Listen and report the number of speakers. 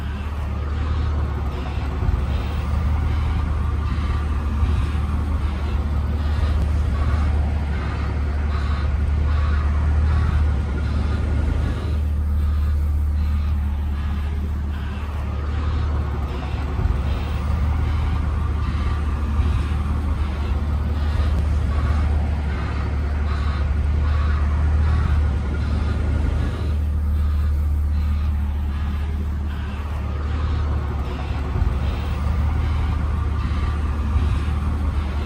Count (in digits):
0